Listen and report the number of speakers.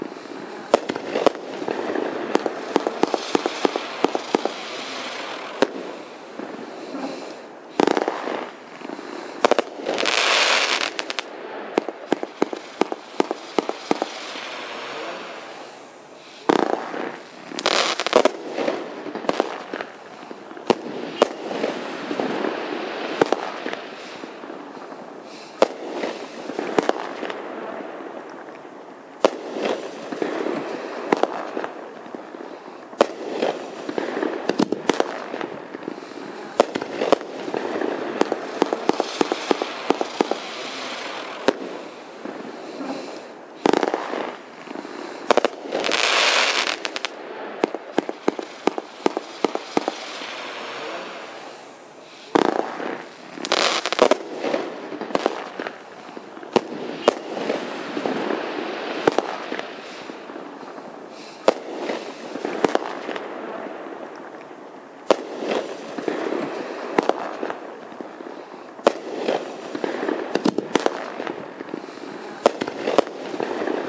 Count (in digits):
0